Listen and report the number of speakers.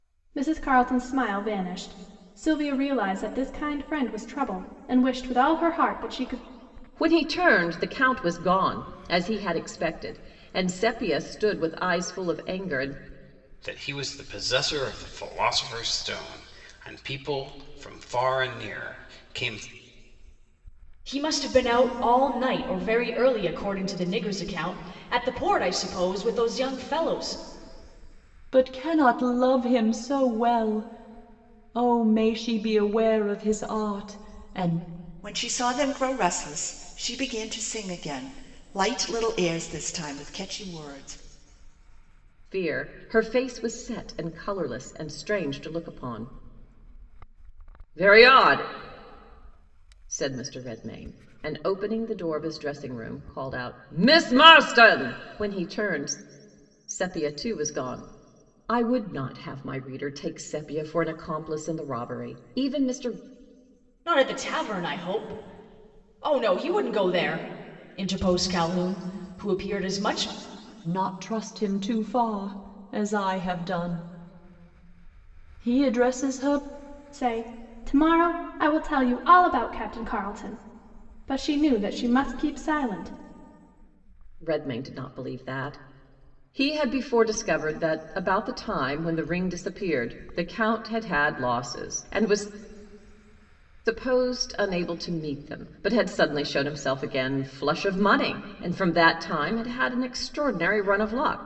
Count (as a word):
six